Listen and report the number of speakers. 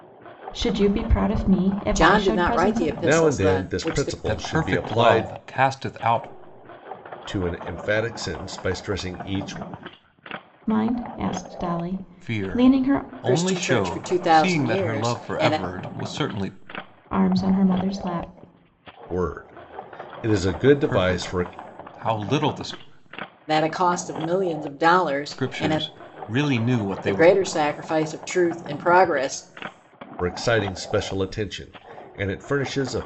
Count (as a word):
four